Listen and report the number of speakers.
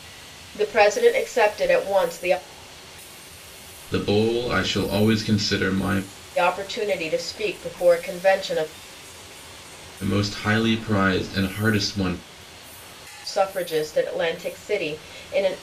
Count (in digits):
2